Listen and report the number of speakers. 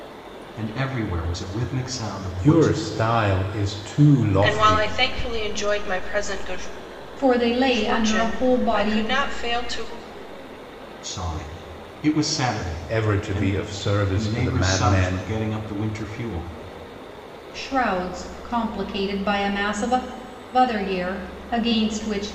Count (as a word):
four